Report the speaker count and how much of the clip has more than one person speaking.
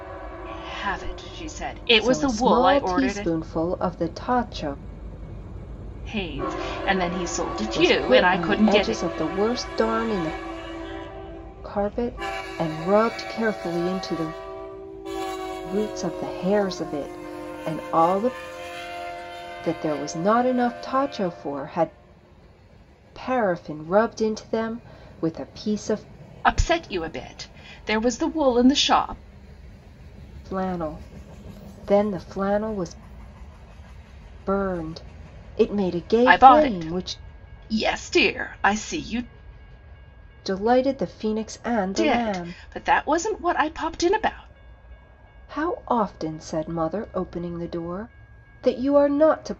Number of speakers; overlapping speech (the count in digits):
2, about 9%